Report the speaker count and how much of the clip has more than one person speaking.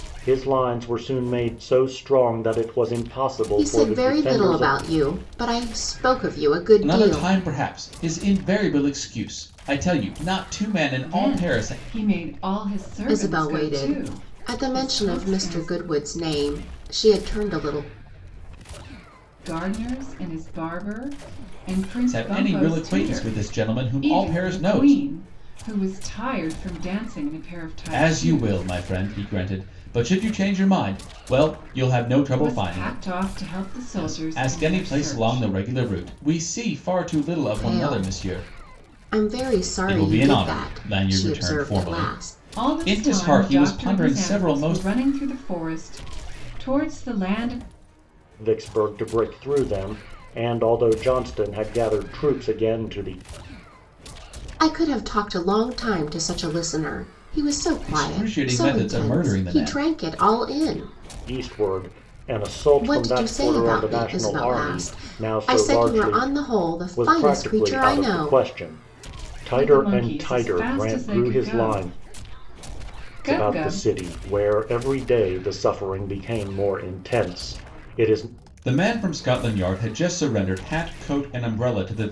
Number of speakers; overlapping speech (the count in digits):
4, about 35%